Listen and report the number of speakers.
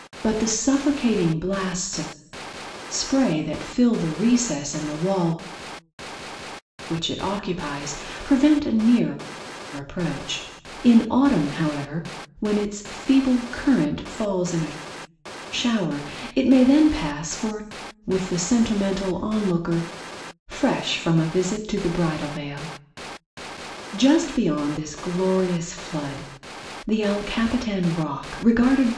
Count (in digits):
1